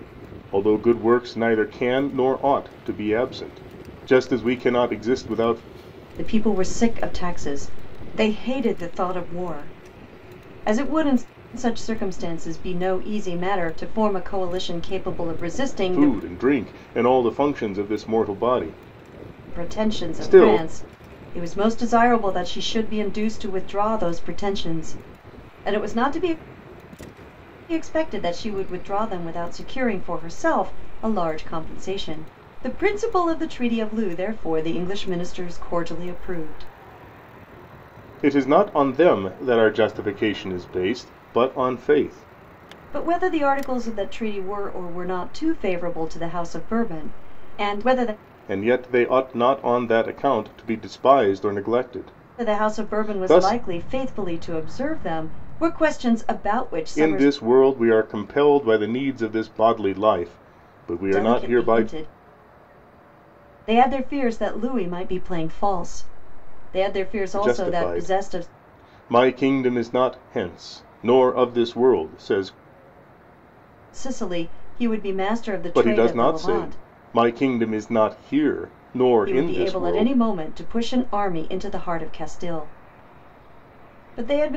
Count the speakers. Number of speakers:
2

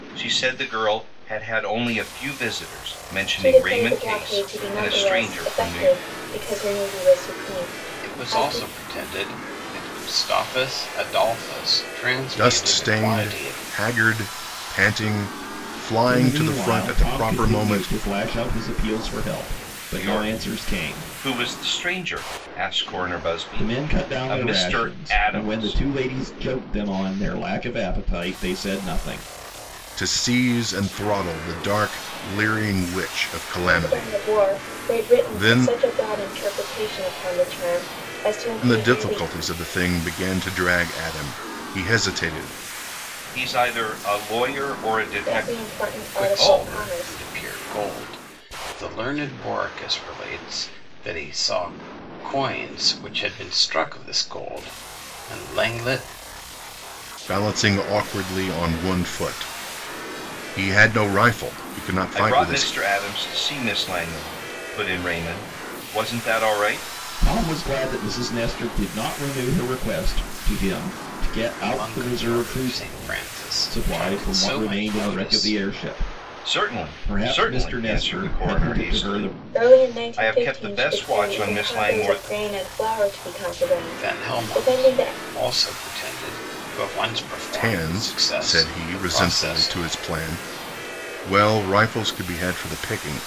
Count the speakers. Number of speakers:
5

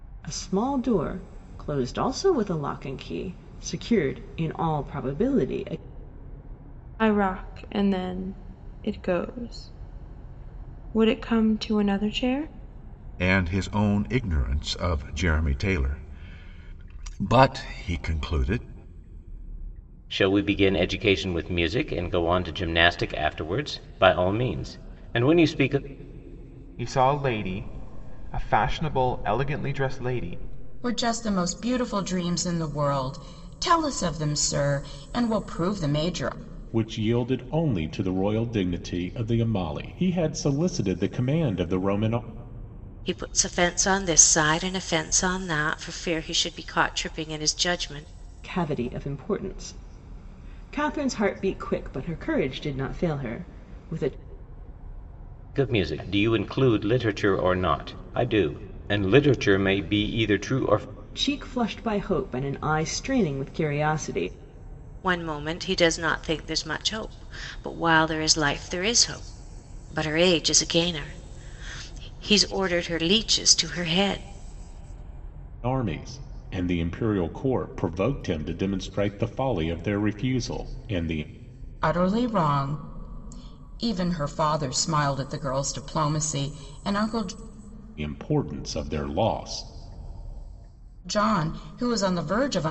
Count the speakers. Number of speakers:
8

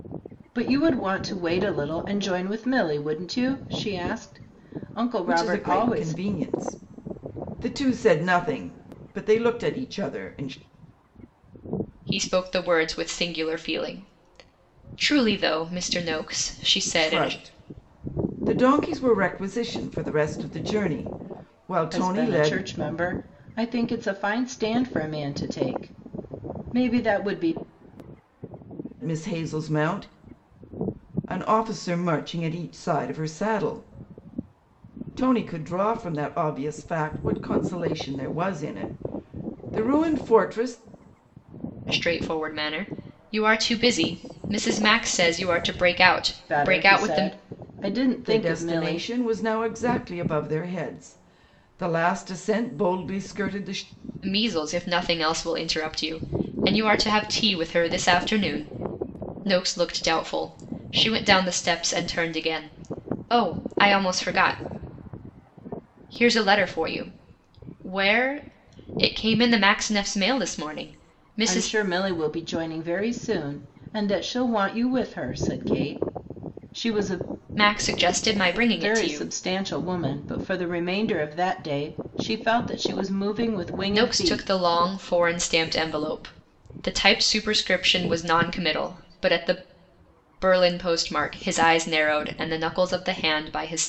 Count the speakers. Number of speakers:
3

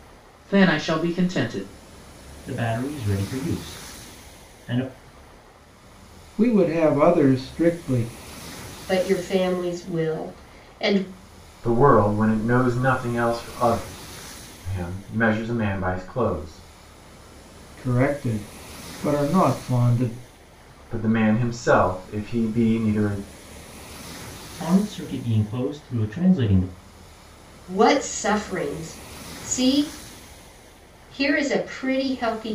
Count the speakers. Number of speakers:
5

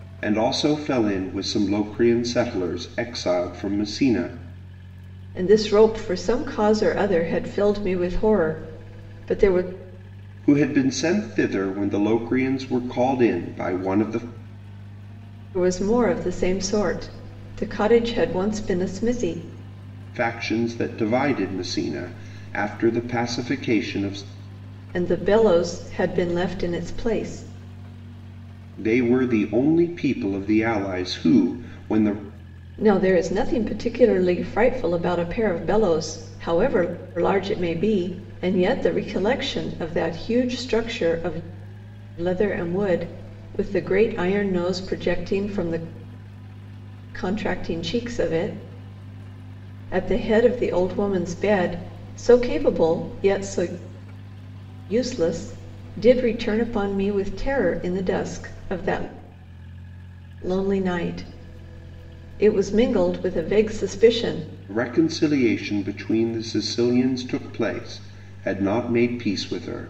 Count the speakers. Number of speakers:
2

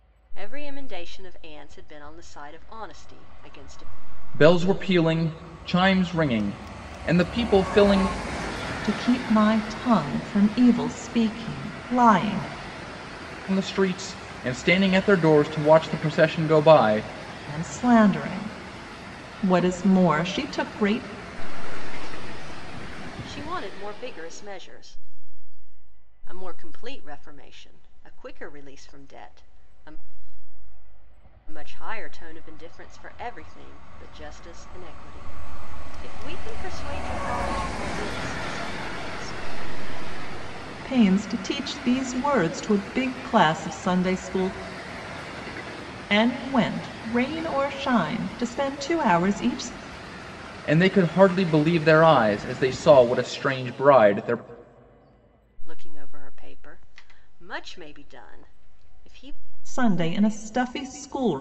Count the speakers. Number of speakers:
3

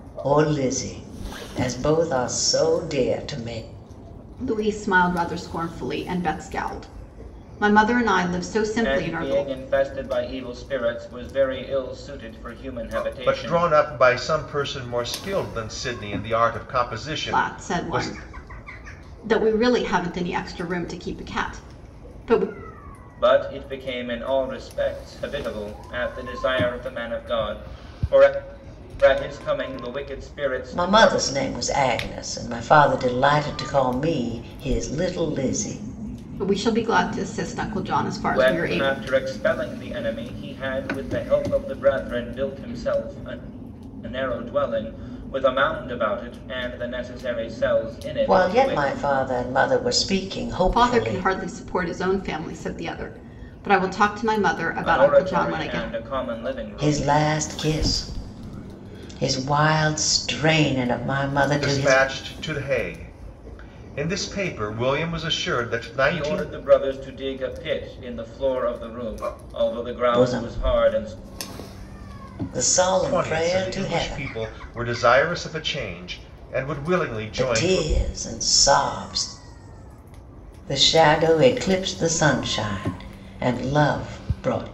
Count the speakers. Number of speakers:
4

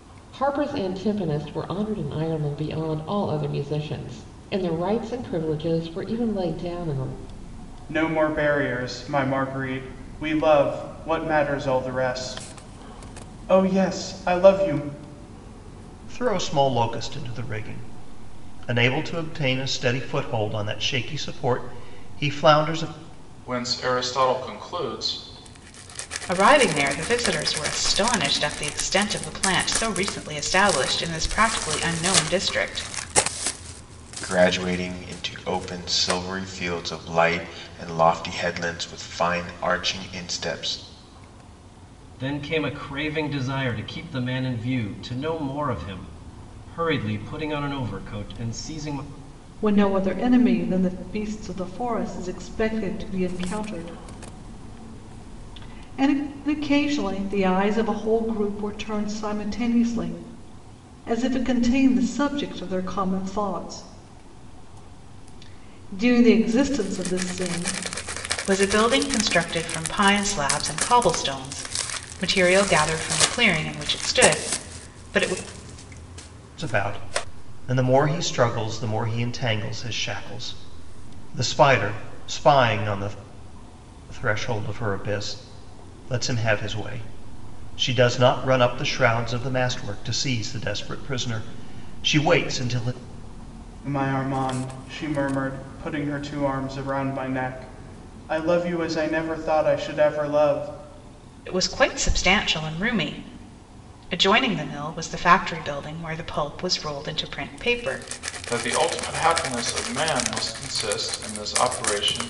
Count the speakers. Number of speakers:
8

